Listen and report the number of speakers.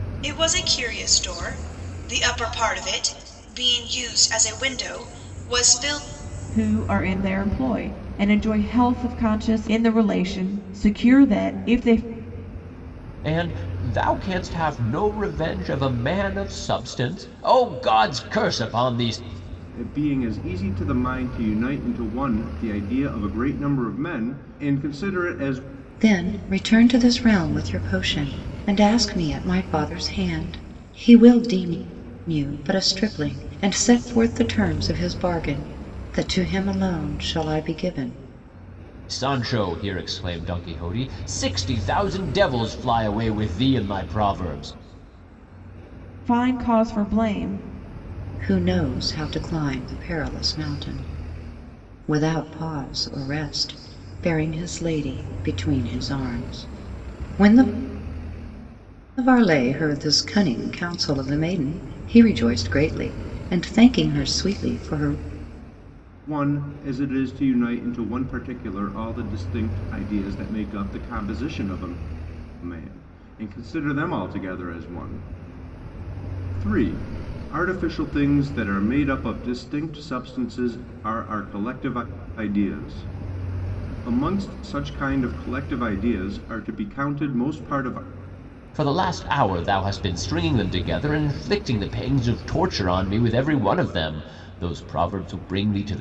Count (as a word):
five